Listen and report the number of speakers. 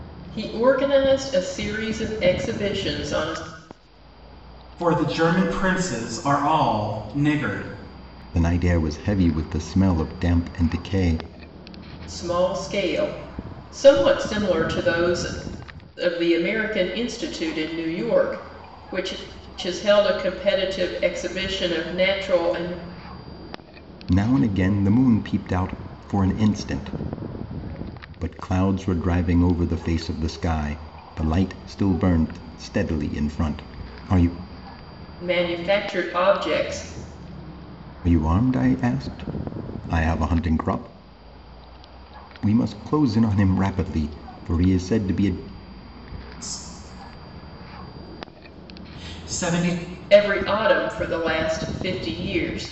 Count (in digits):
3